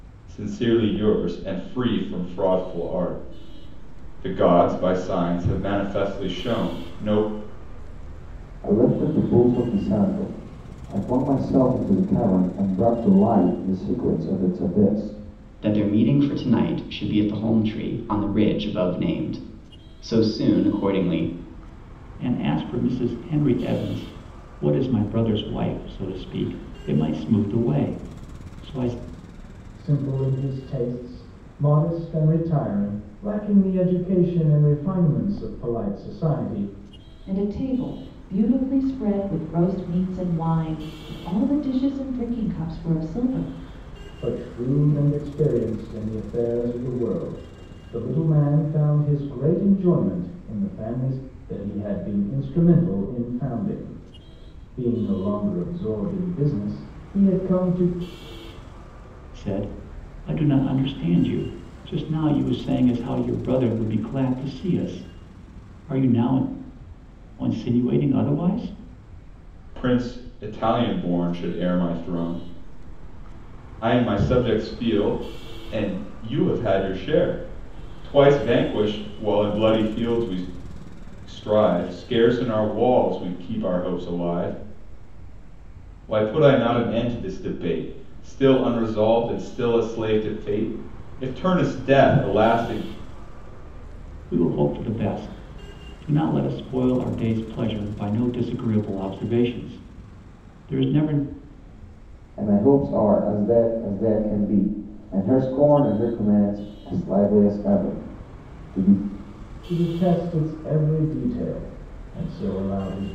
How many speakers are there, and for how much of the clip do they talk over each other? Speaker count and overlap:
6, no overlap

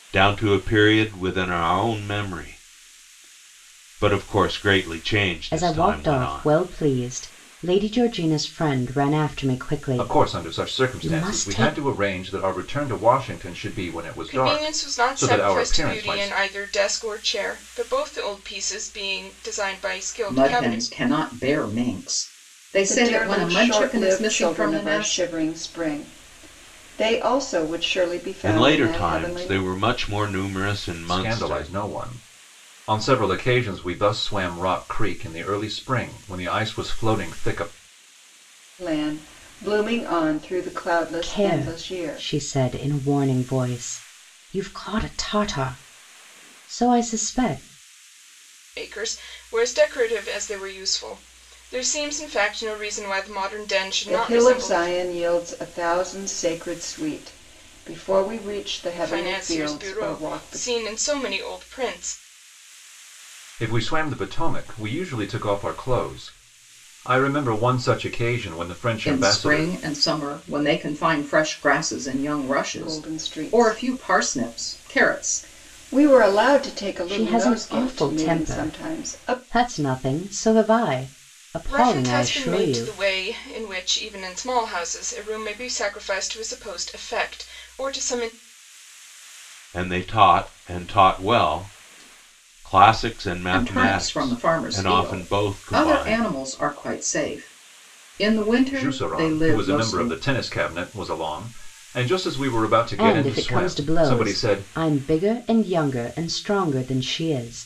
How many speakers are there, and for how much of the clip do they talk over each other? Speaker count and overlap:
6, about 25%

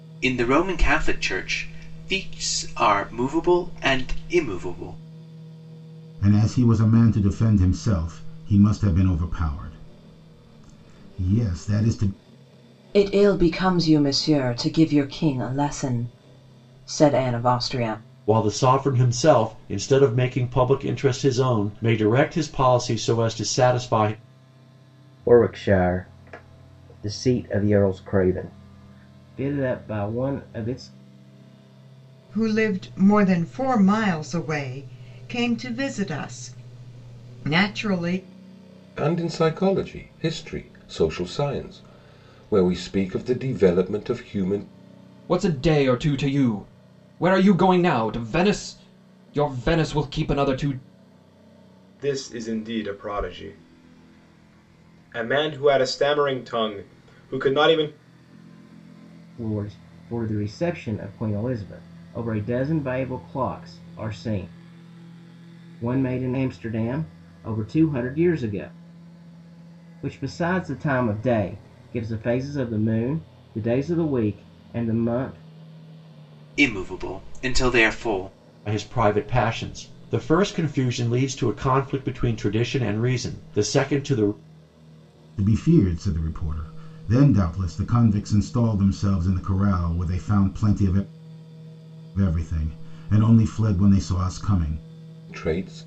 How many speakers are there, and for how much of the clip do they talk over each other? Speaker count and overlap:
9, no overlap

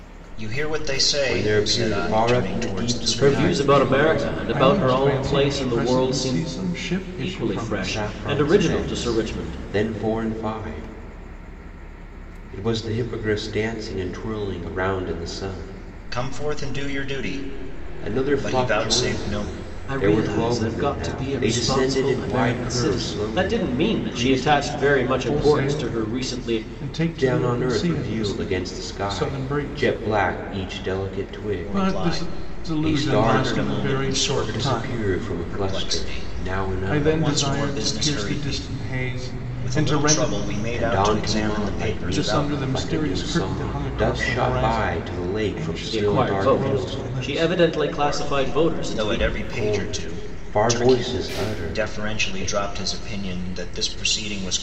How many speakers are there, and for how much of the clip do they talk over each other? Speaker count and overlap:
4, about 66%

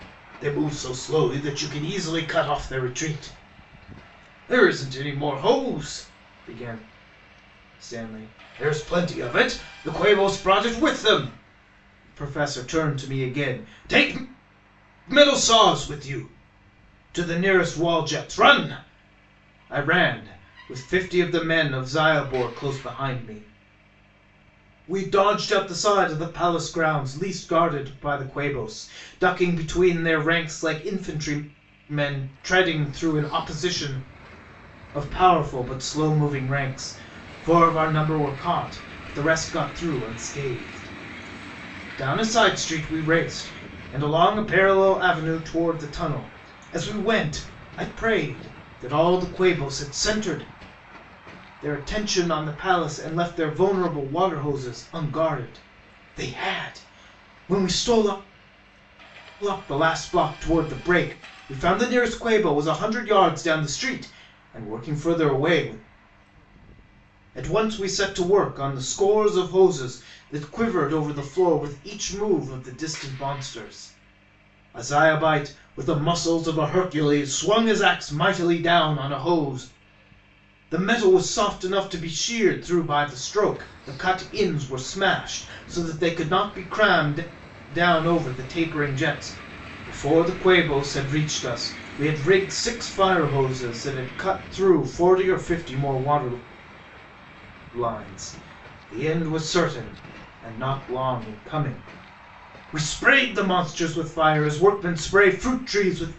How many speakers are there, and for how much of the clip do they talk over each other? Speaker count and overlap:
1, no overlap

